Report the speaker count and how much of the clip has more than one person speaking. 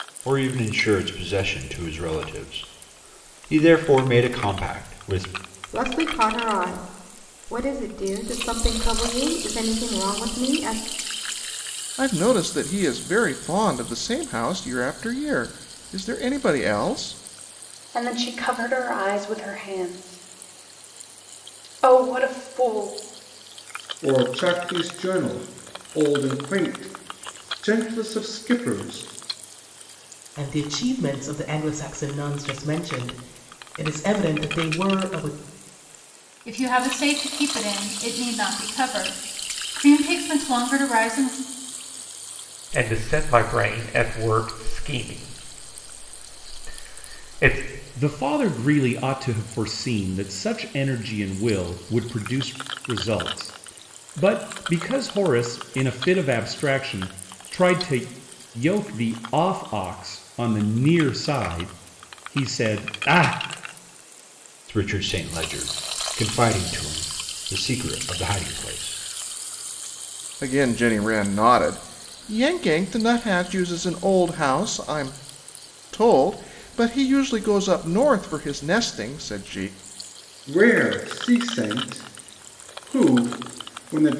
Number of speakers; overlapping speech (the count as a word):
nine, no overlap